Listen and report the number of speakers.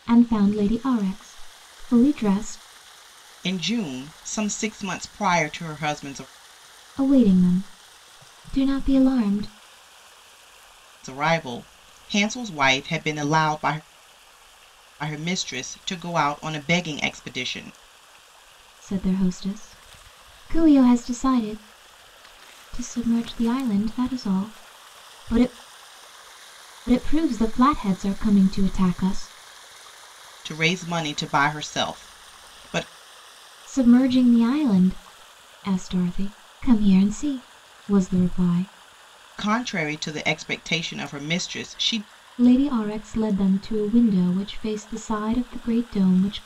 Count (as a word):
two